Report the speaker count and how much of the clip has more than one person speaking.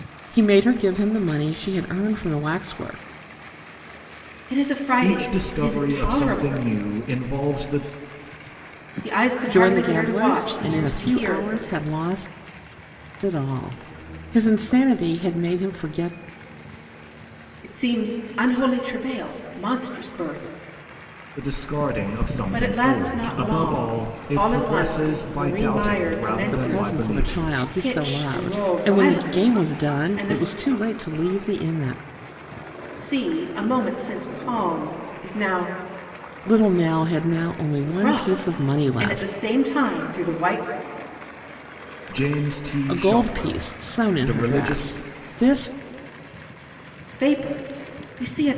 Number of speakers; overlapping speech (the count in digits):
3, about 31%